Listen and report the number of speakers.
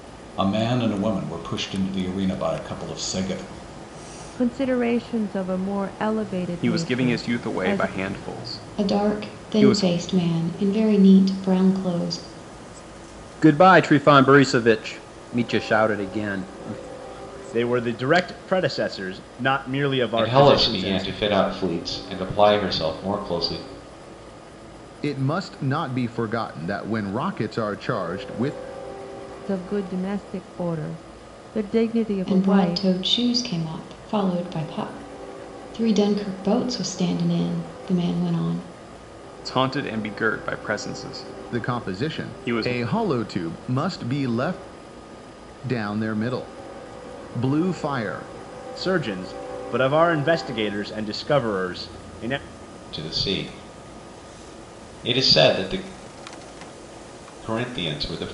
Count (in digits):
8